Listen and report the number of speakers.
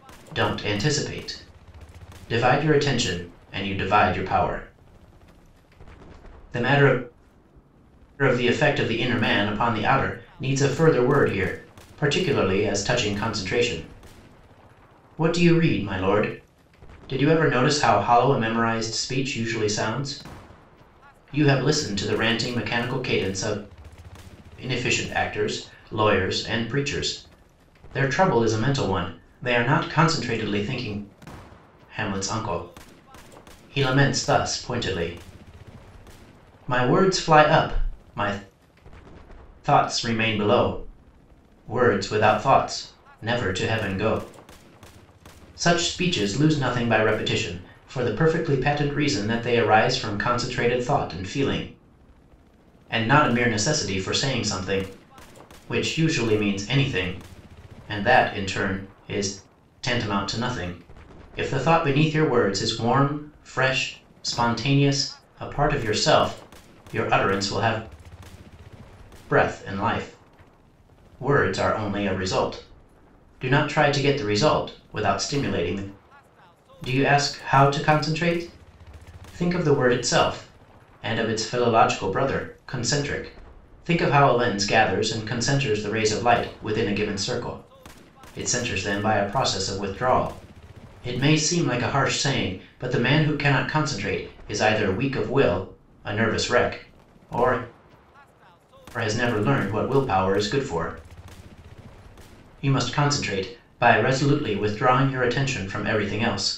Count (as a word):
one